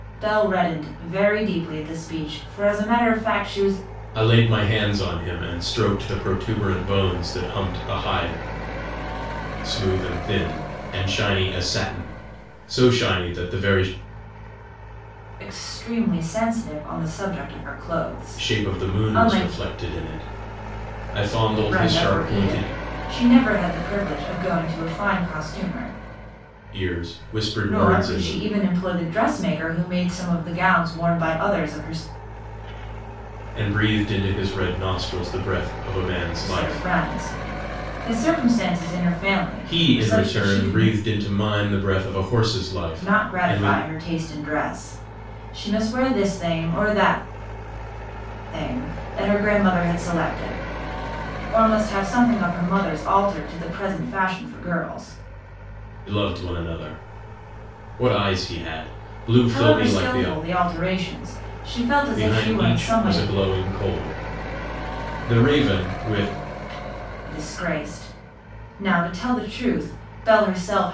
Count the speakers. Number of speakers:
2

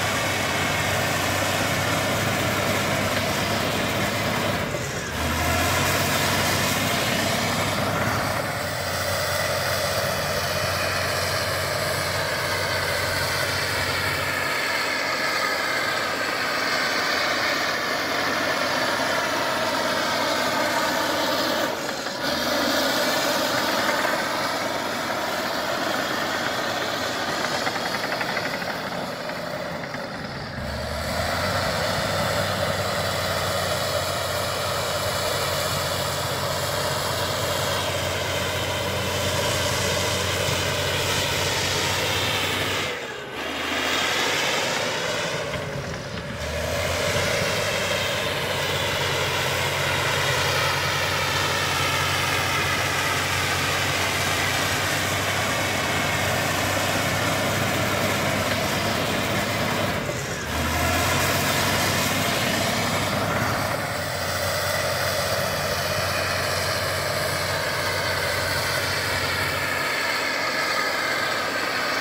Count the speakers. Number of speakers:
0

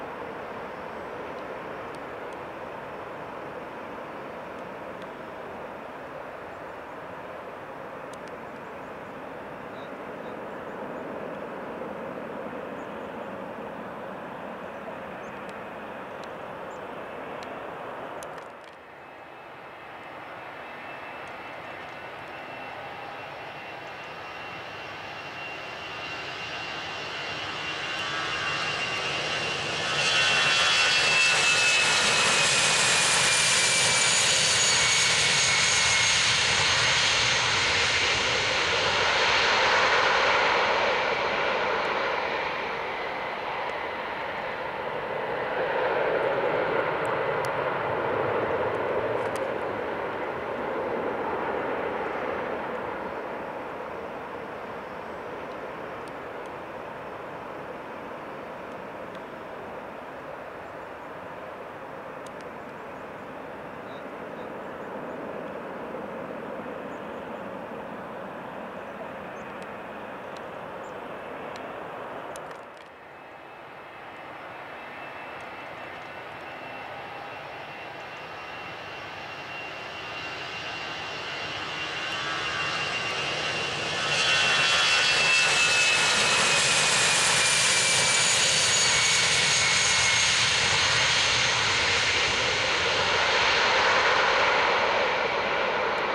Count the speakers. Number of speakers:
0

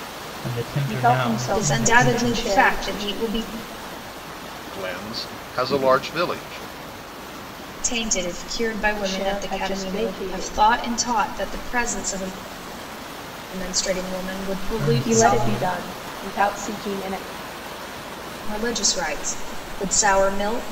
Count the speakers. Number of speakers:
4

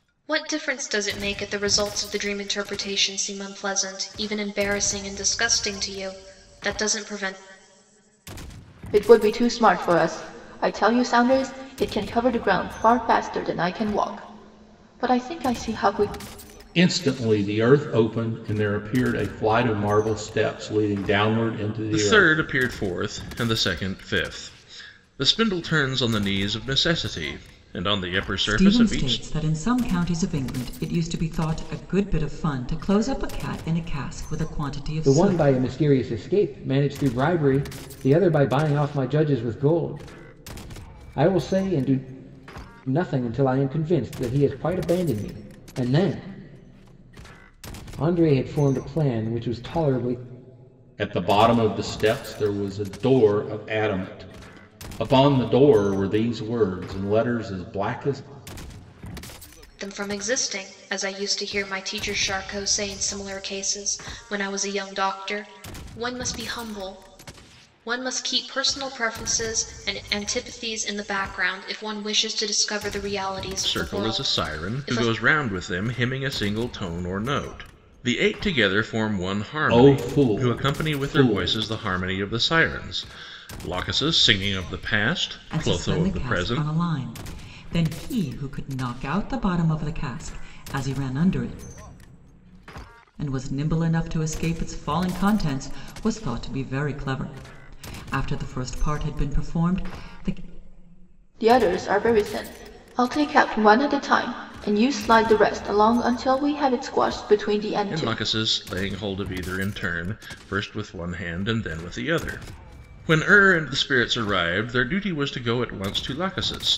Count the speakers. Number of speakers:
6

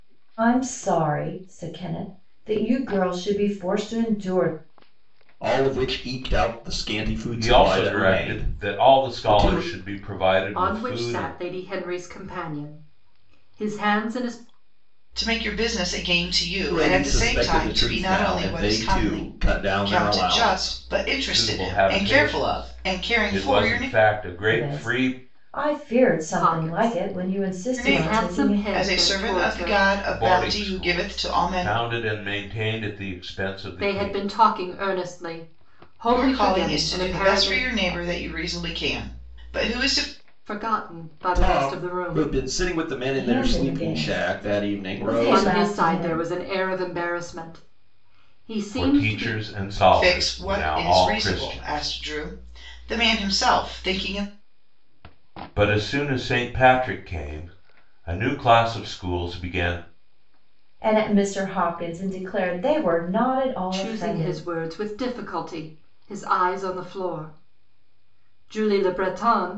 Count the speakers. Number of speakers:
5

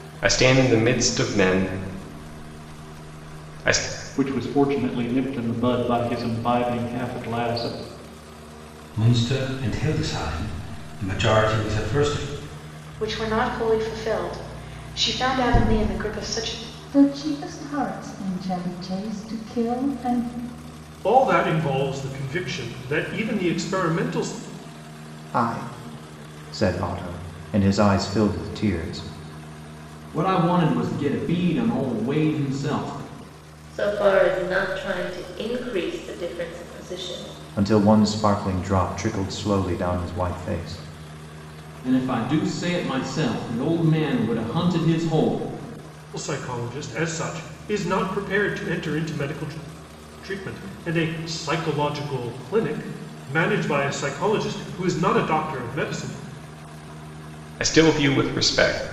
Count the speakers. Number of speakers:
9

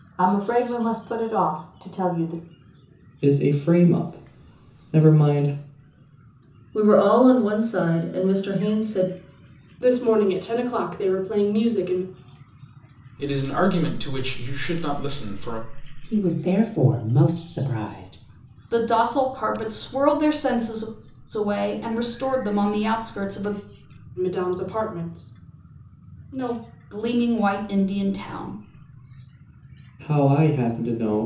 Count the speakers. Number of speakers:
7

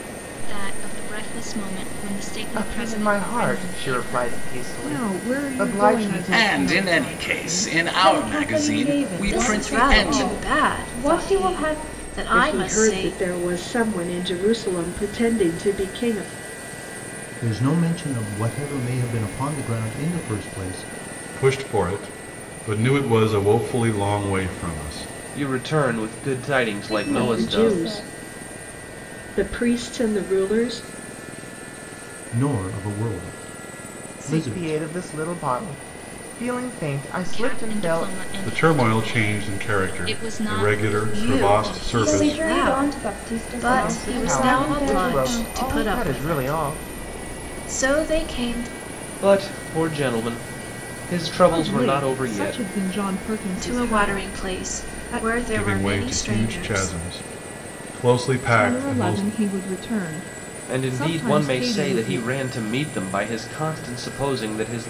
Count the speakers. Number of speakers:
10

